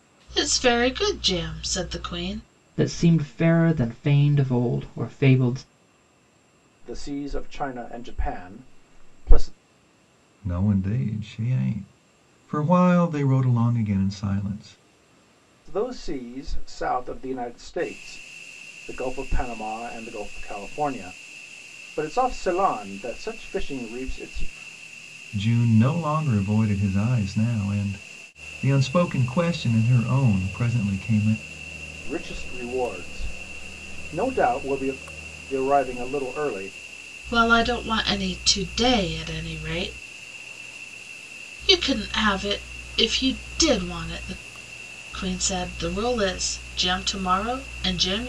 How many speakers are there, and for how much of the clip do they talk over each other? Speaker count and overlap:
4, no overlap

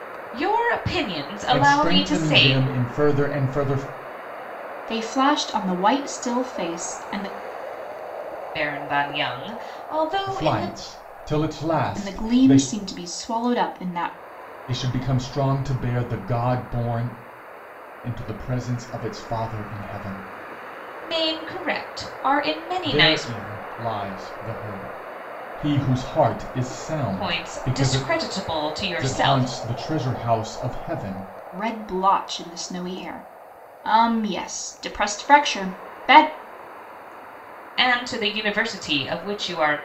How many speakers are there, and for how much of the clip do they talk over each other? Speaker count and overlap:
3, about 11%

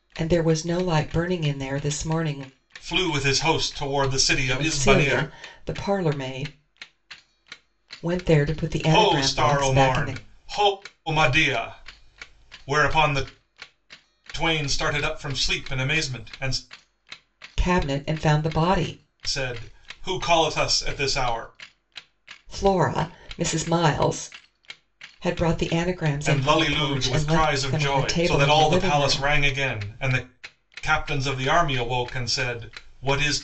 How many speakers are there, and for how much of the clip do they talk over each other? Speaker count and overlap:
2, about 16%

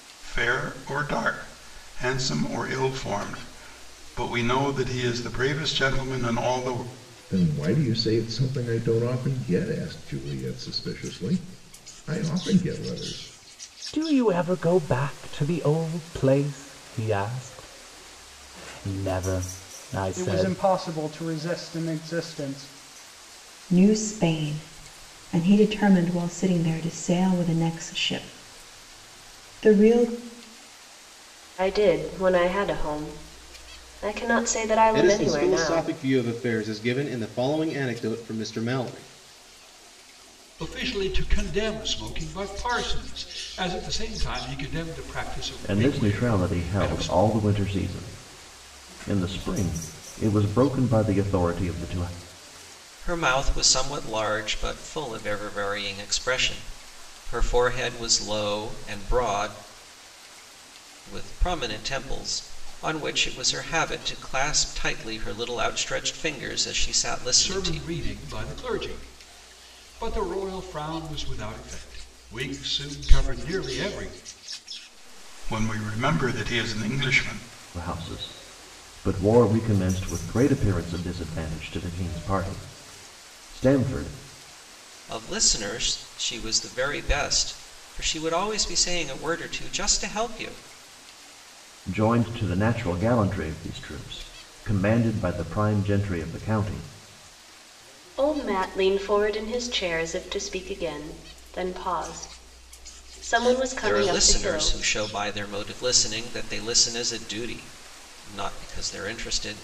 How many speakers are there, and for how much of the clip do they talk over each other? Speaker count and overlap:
10, about 4%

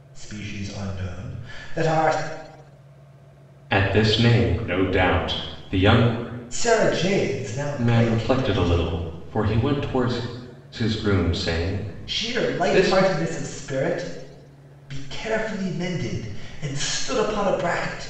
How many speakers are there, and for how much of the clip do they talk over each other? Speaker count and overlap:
2, about 10%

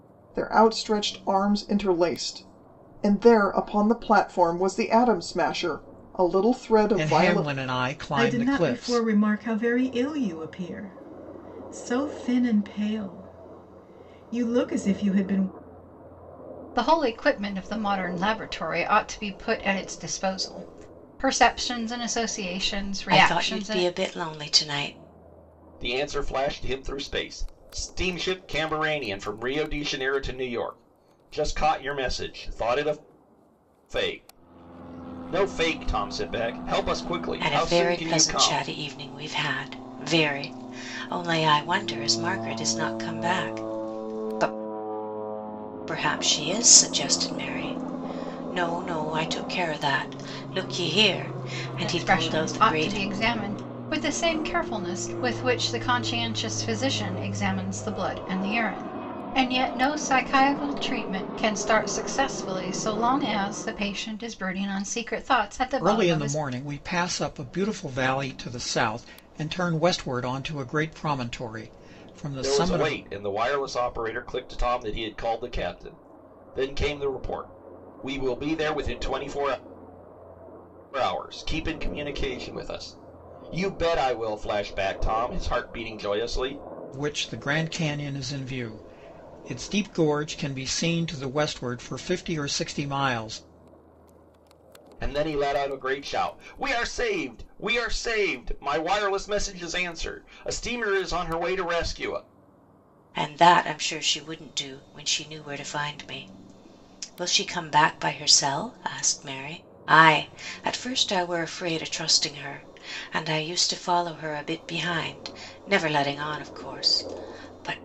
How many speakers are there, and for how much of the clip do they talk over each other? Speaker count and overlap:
6, about 5%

